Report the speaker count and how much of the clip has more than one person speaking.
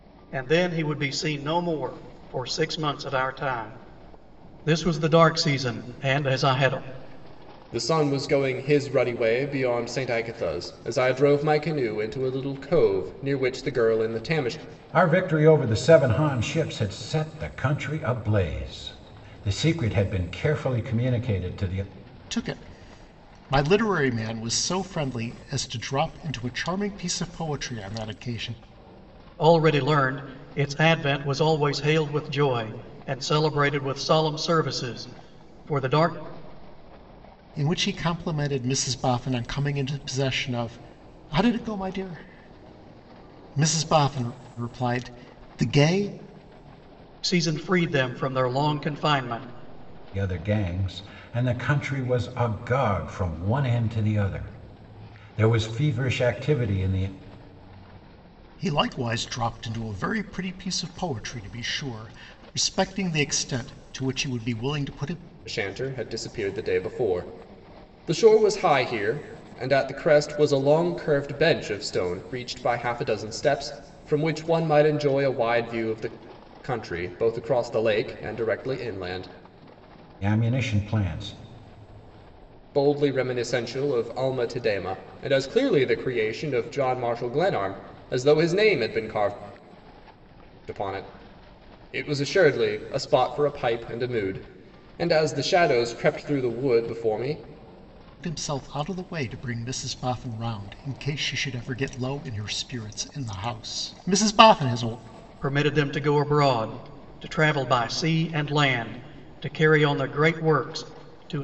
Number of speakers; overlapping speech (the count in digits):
4, no overlap